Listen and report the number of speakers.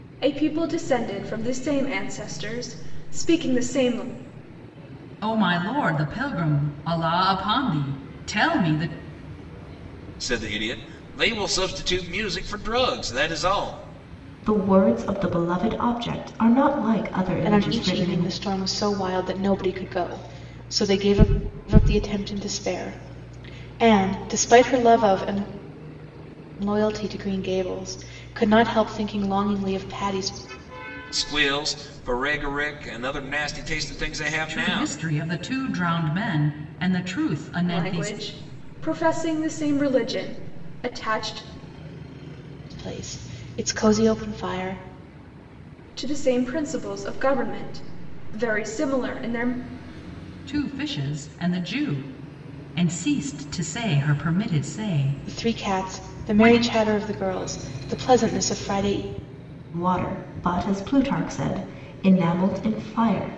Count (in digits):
5